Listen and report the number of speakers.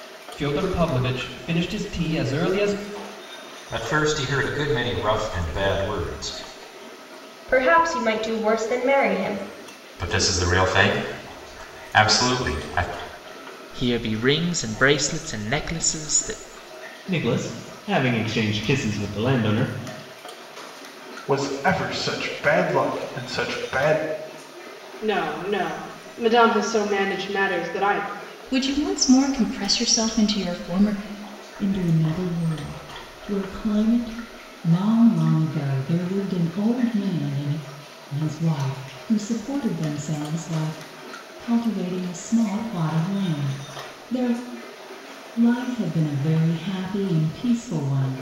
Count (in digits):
10